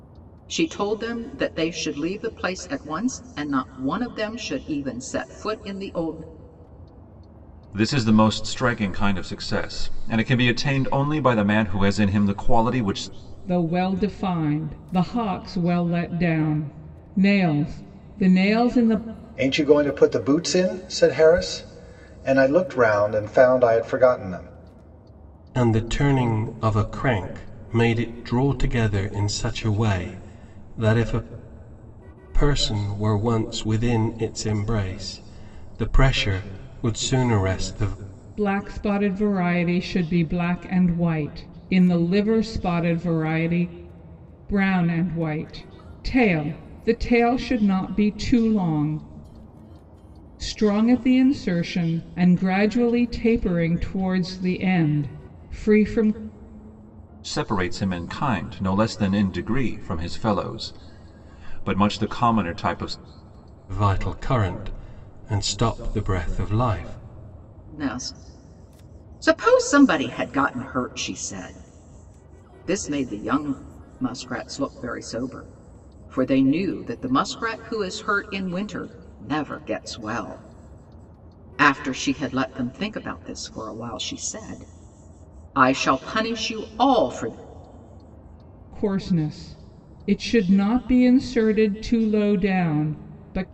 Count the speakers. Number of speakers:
5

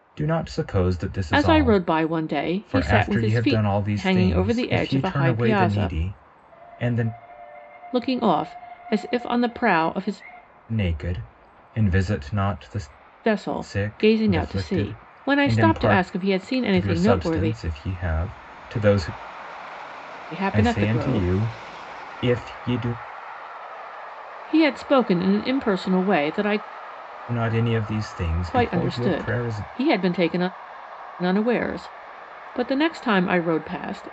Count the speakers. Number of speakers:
2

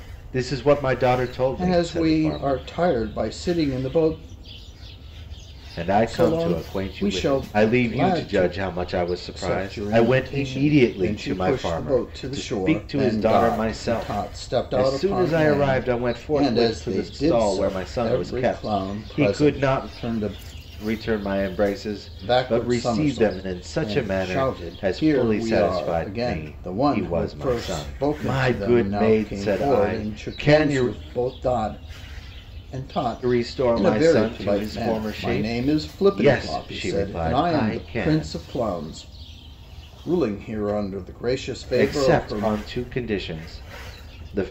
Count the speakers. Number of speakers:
2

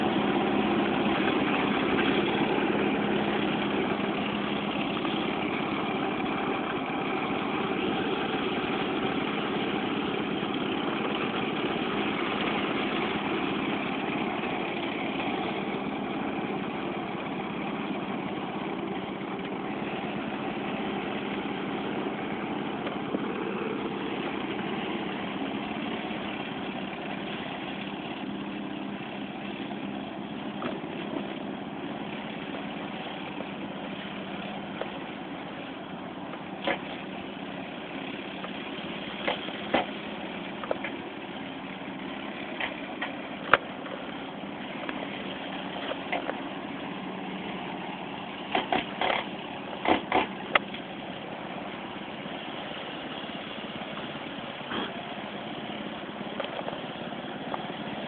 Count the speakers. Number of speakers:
0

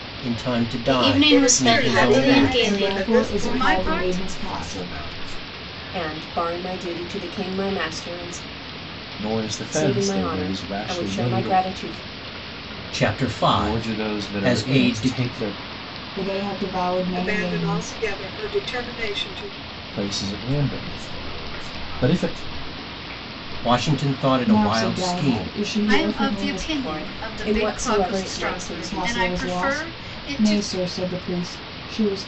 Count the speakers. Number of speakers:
8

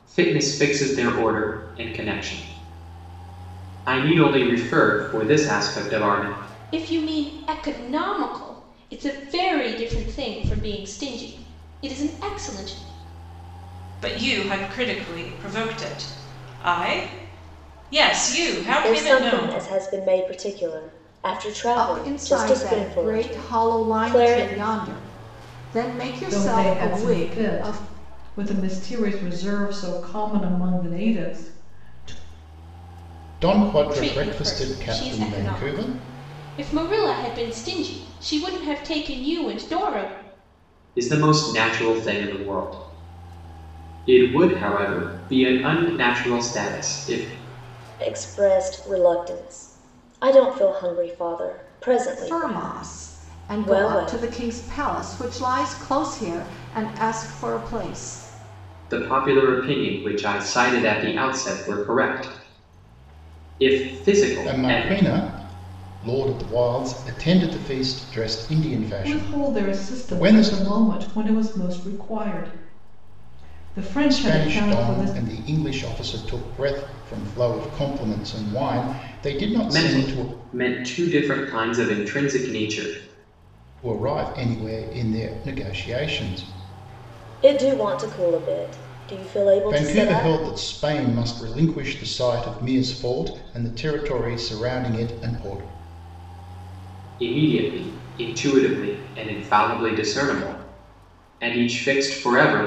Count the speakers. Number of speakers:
7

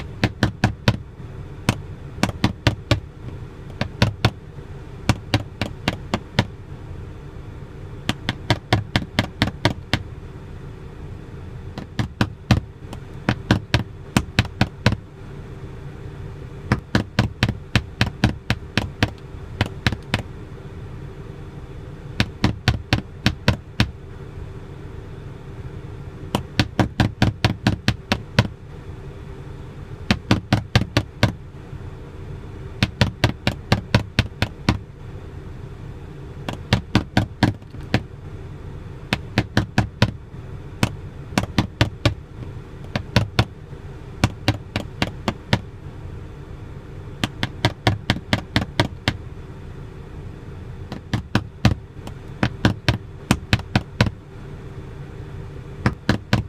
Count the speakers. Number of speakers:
0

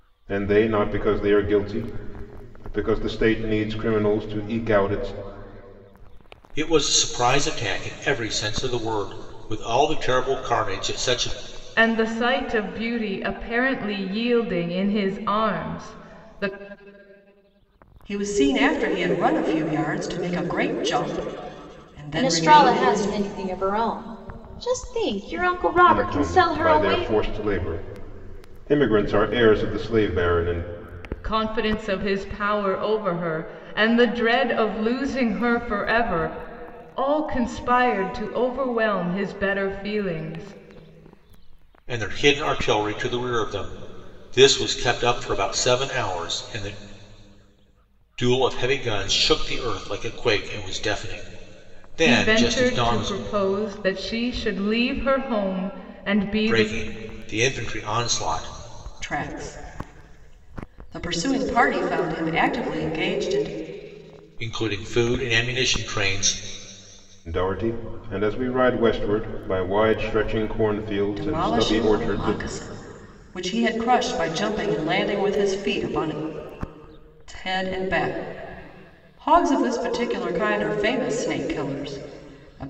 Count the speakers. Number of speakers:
5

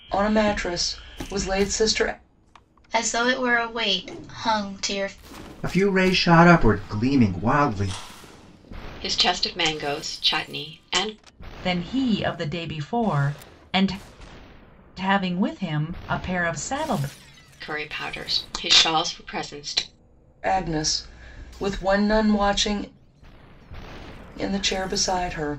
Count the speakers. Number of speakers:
5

